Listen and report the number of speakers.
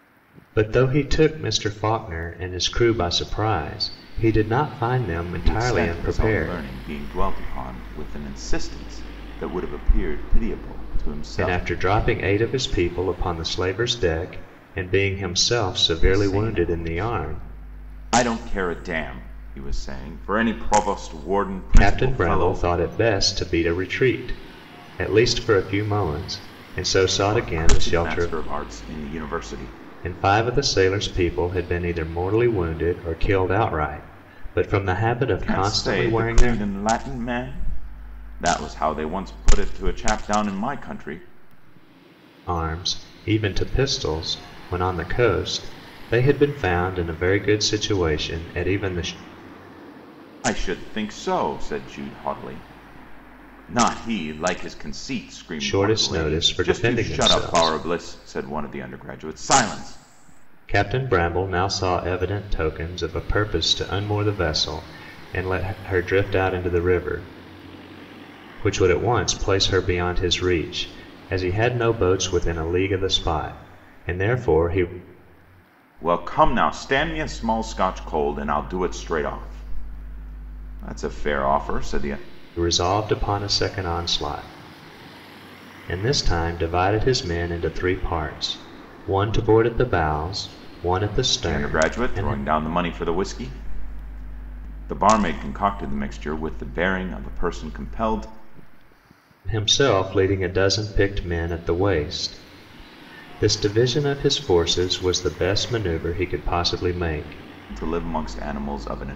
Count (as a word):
two